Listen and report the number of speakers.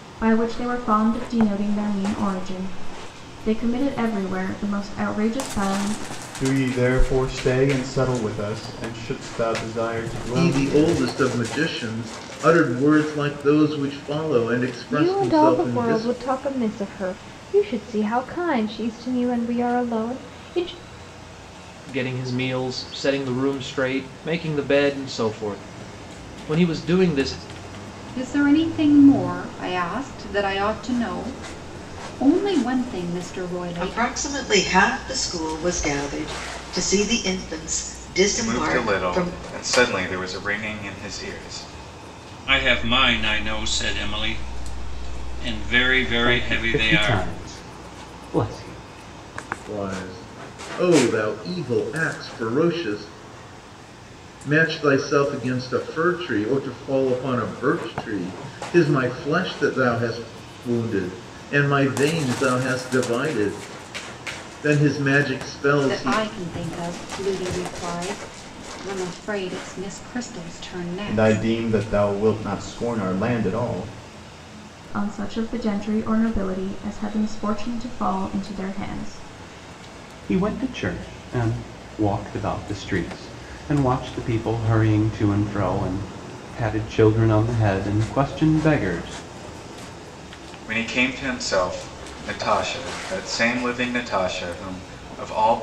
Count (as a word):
ten